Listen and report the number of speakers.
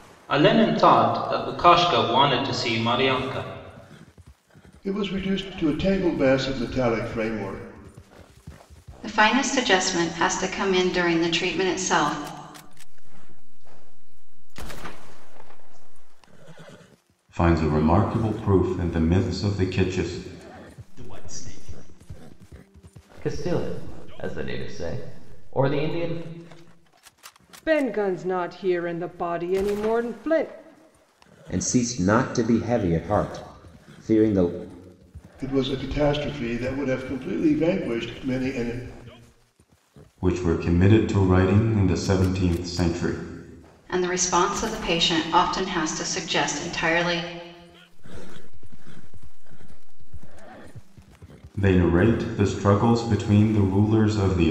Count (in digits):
9